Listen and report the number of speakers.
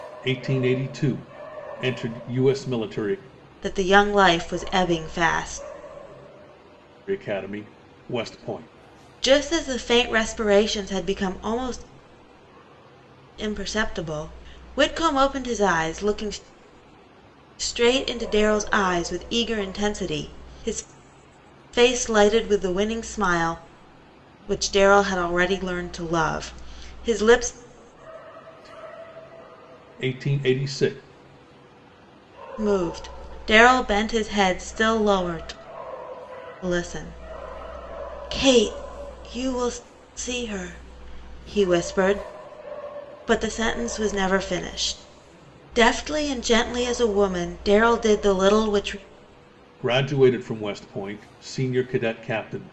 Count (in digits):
2